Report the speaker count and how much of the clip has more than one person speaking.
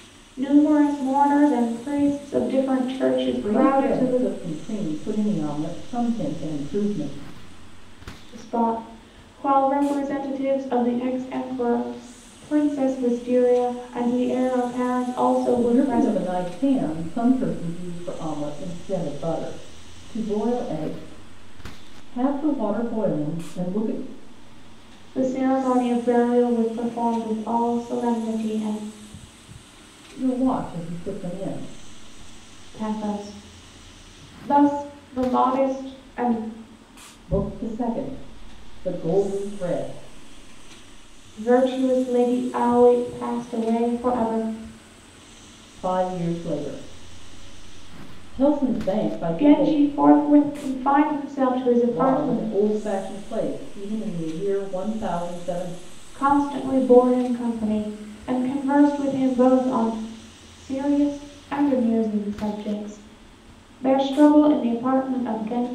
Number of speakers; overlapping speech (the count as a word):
two, about 4%